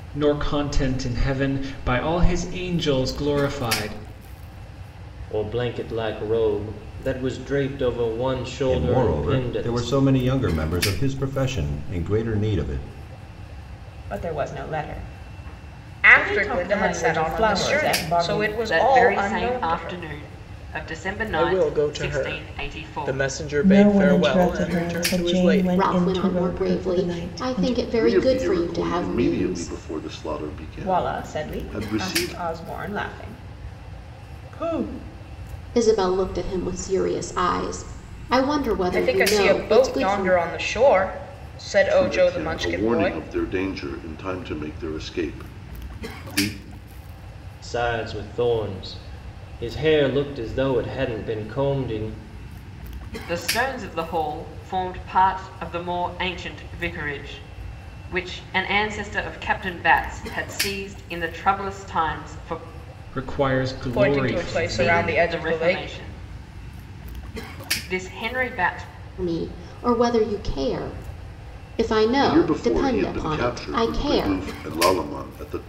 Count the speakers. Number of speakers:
10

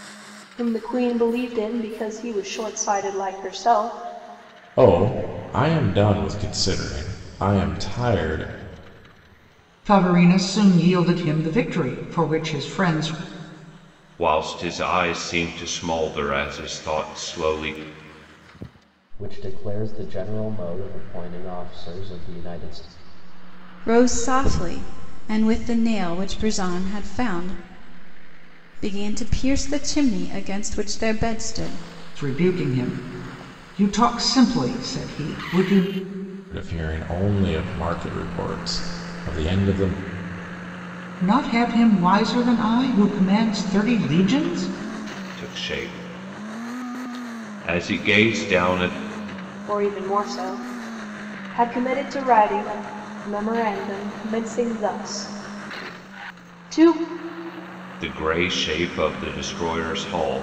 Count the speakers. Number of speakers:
6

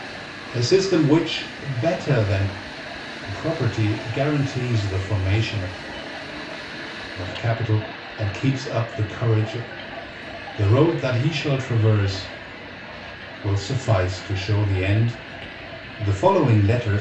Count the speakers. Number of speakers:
1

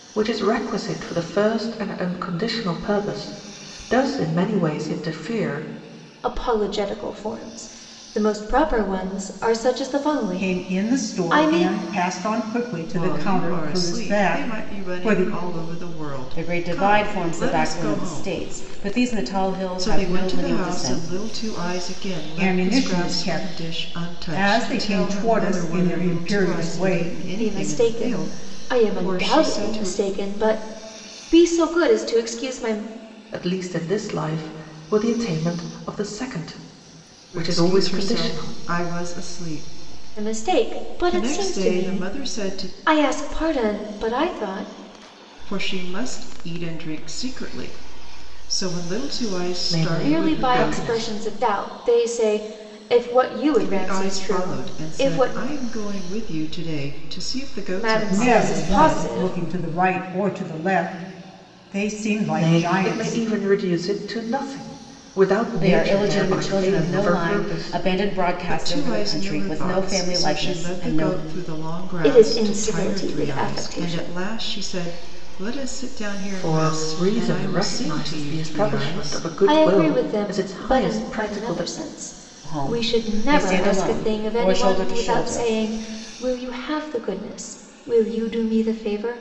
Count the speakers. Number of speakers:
5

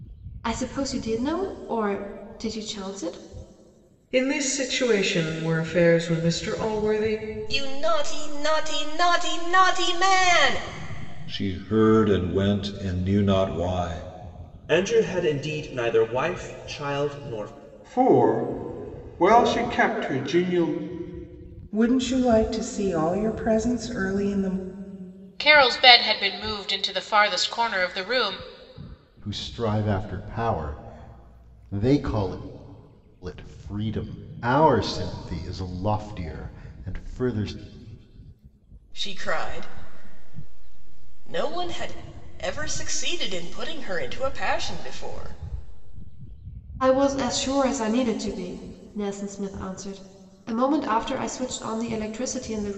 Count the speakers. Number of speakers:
9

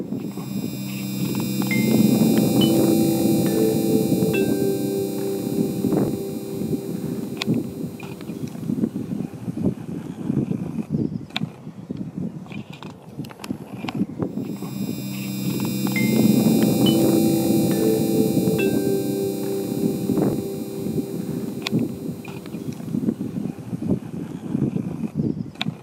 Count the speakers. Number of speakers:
0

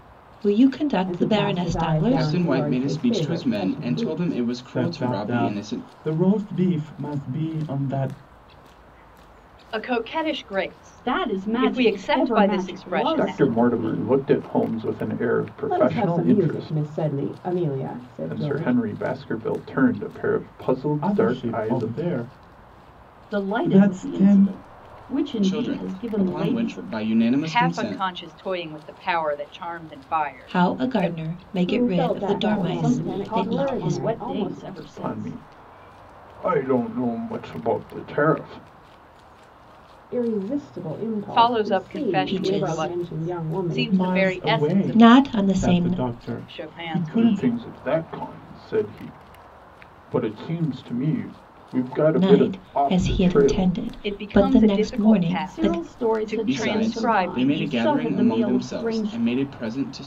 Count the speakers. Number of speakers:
7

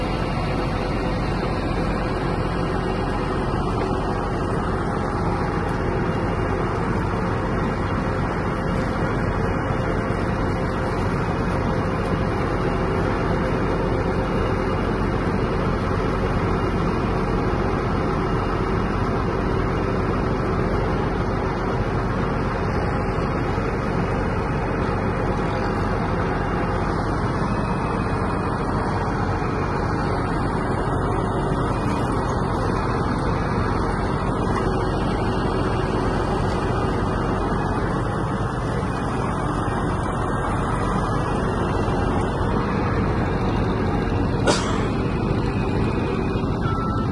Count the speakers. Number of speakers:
0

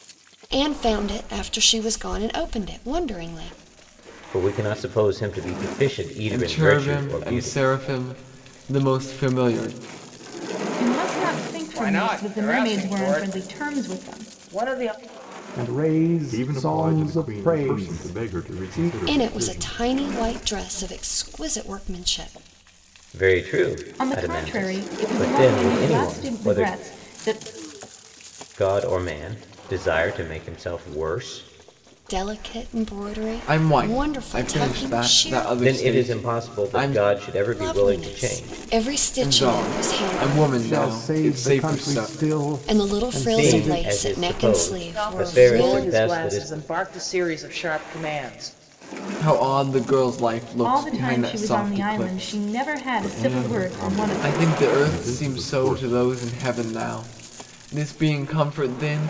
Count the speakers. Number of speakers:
7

